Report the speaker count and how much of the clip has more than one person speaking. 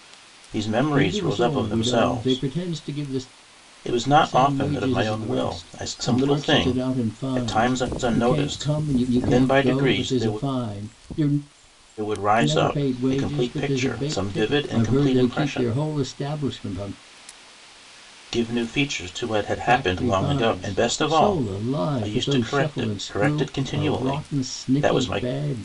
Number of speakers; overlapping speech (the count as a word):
two, about 63%